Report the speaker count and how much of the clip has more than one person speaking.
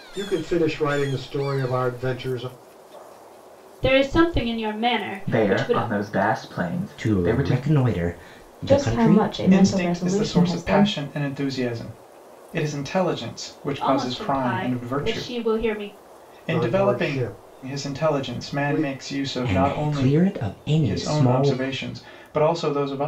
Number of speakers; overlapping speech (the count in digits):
6, about 39%